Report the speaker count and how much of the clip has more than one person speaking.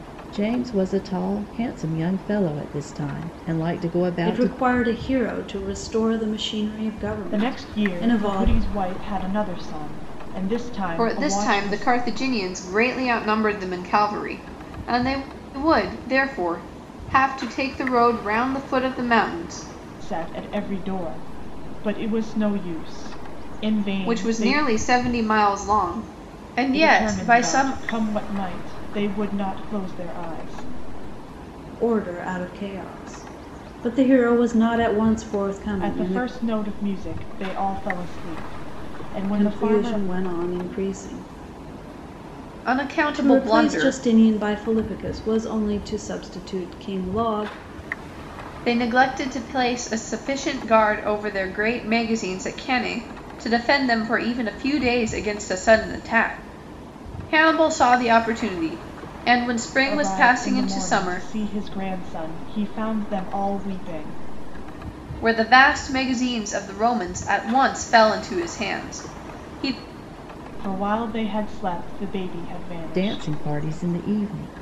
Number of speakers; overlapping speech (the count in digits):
4, about 11%